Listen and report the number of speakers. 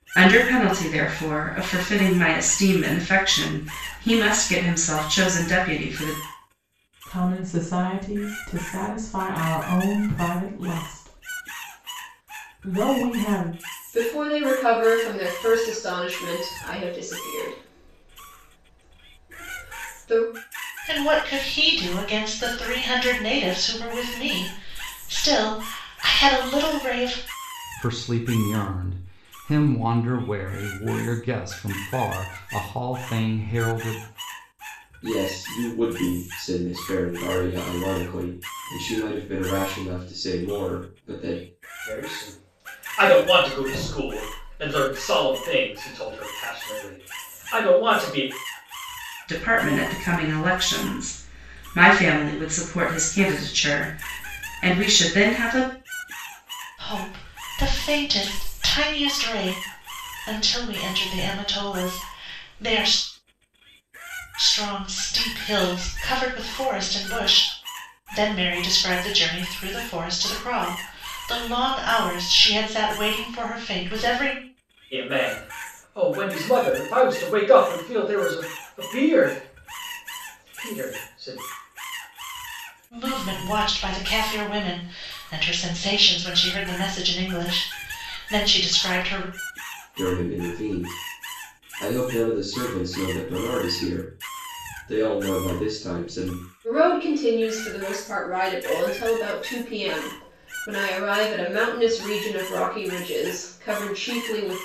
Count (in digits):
7